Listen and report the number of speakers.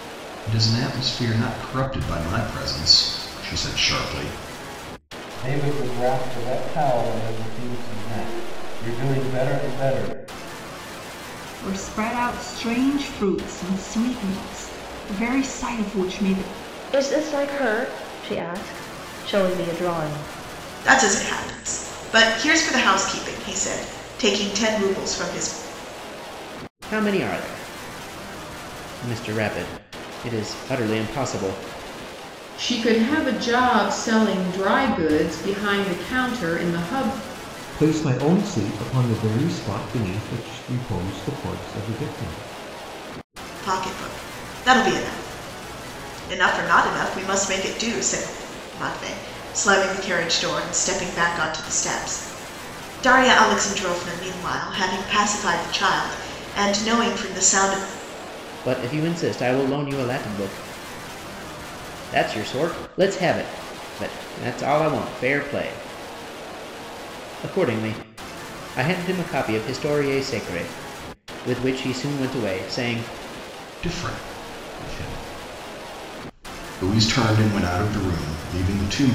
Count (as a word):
eight